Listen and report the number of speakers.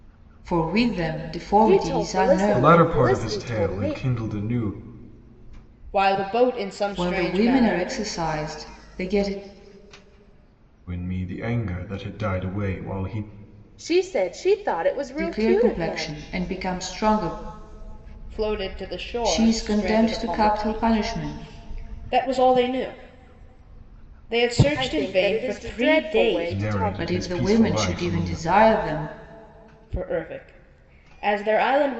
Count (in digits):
4